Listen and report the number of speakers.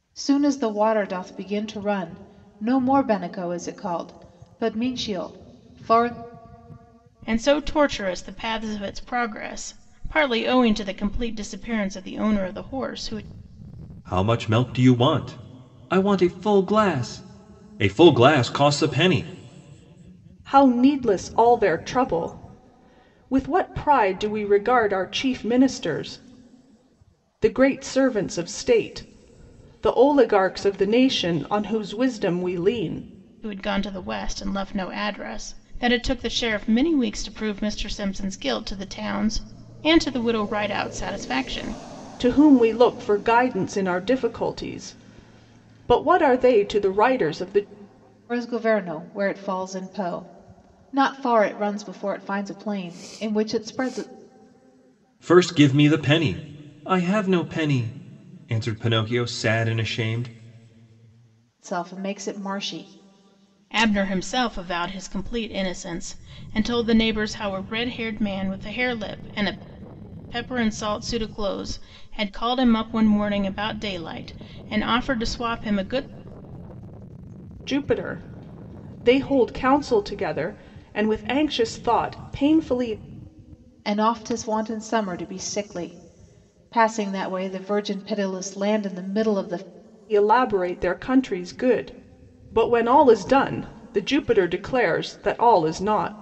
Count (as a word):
four